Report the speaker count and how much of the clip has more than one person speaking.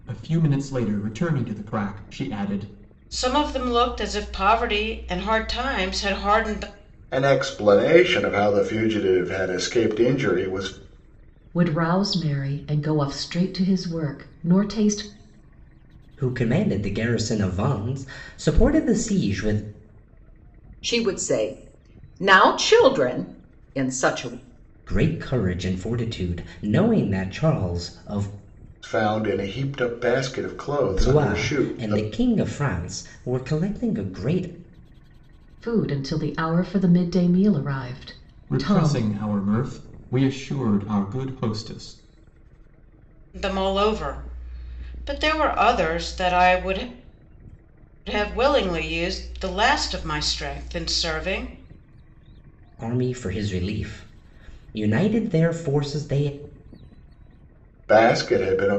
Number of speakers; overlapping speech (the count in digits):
6, about 3%